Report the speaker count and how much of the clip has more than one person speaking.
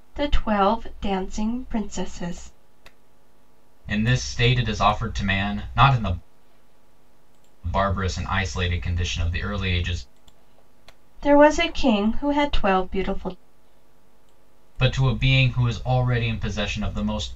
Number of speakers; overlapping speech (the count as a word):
two, no overlap